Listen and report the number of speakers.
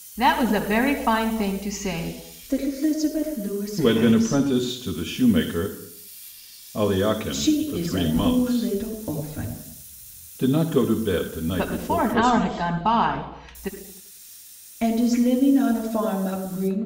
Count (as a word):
three